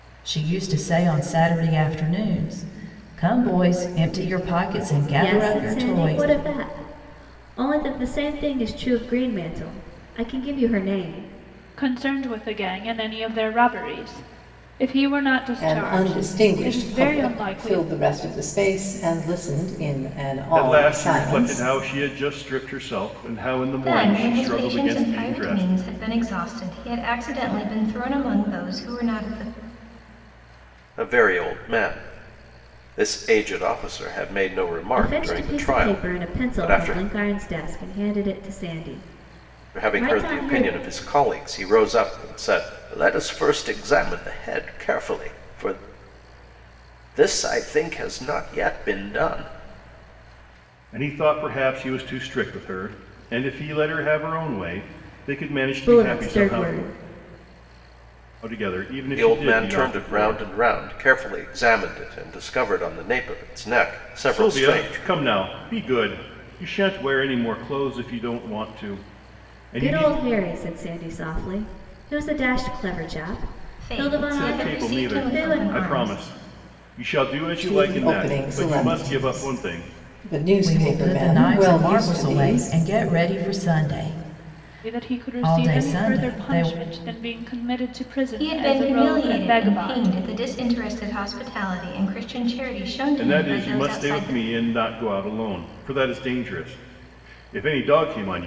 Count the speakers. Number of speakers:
seven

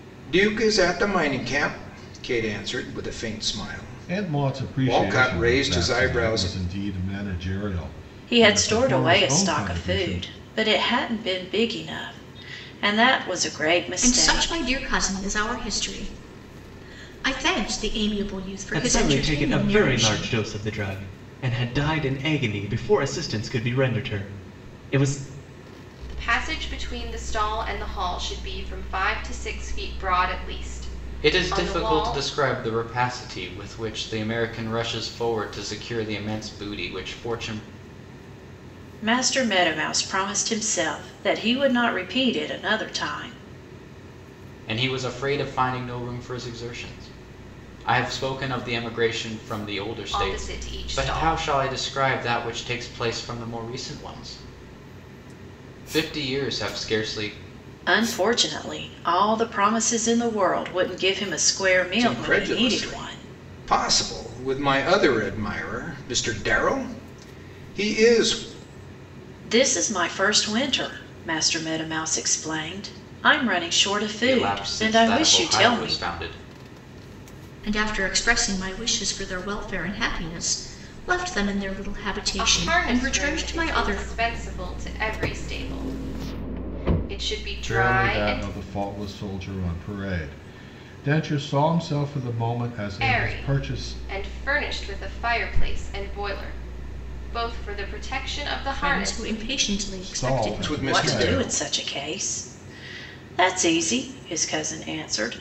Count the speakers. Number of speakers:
seven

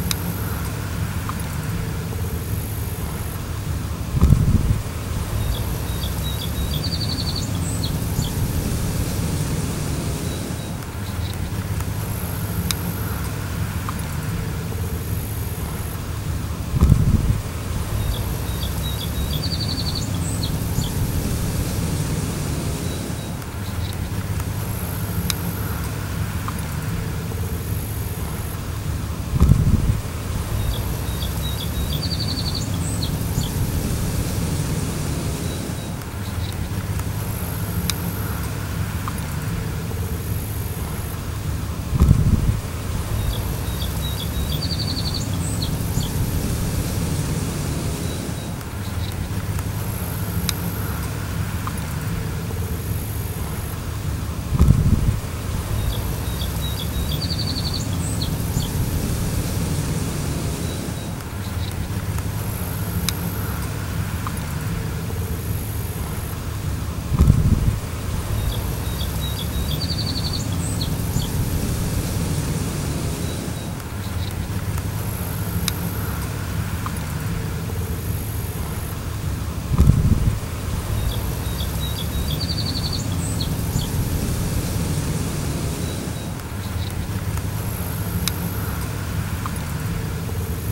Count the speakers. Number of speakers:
zero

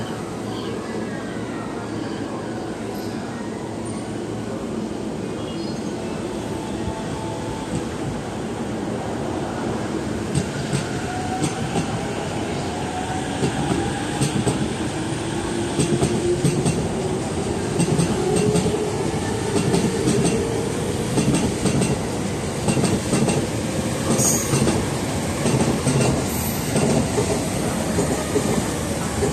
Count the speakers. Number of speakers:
zero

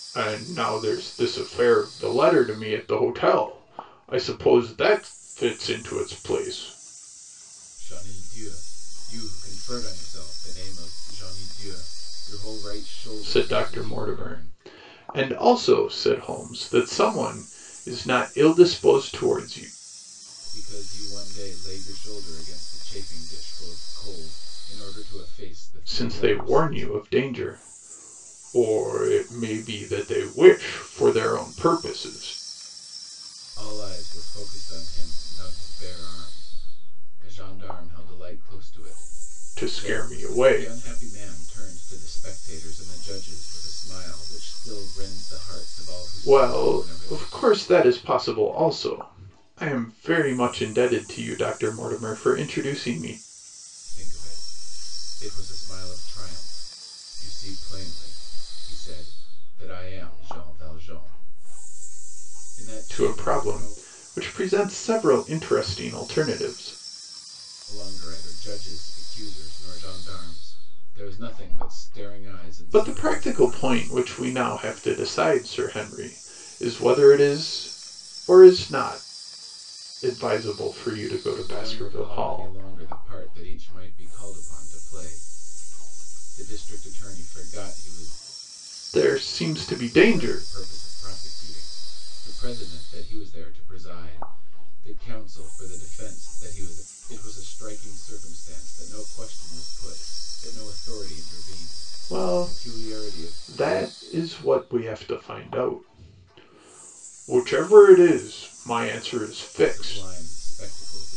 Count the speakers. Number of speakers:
two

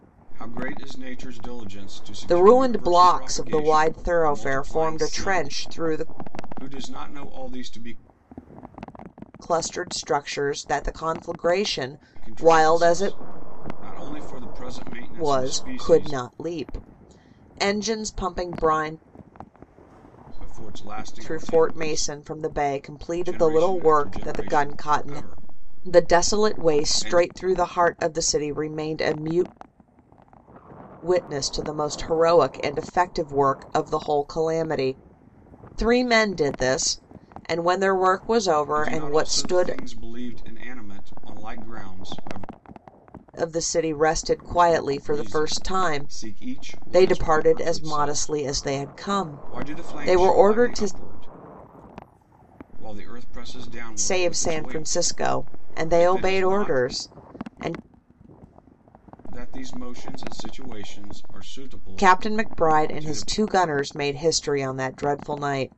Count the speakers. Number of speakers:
two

